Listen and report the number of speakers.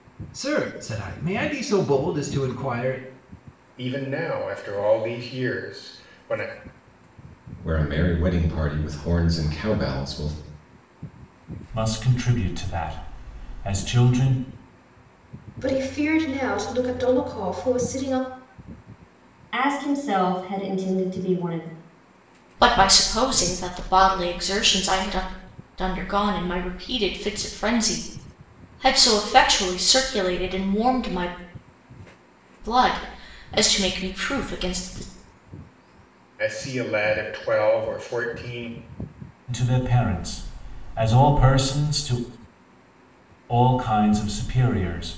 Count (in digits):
7